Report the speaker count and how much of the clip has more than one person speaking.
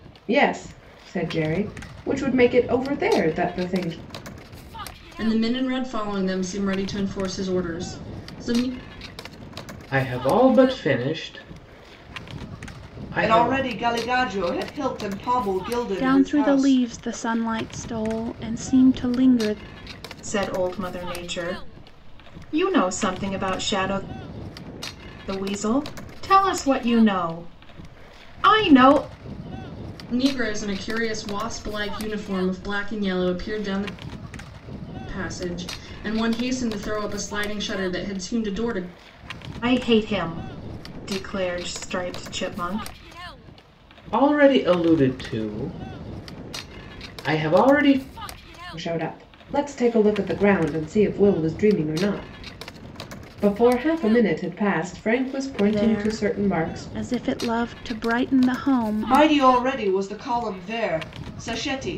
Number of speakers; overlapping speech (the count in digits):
6, about 5%